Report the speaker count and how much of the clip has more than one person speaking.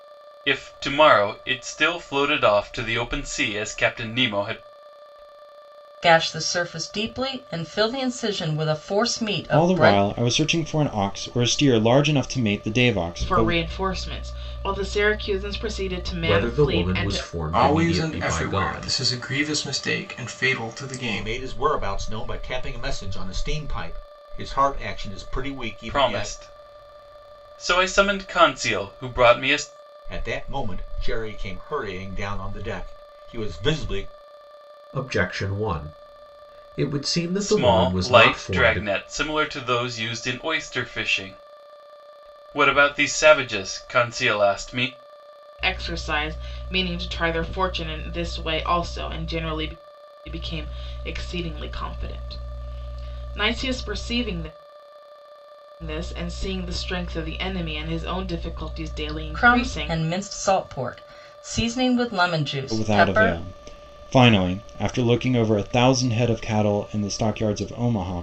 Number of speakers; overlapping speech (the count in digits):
7, about 11%